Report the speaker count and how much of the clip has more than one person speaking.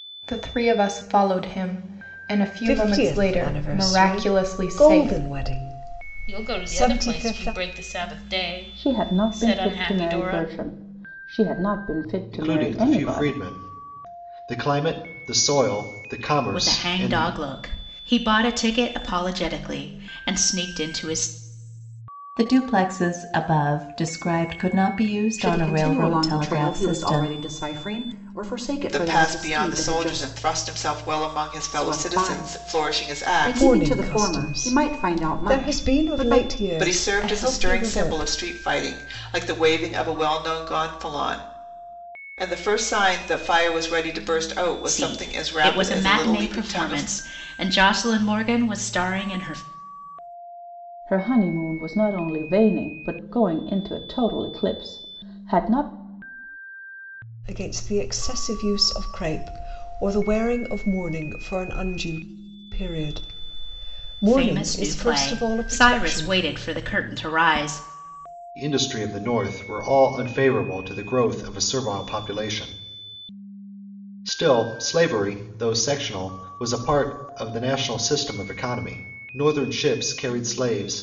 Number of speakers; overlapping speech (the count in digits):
9, about 27%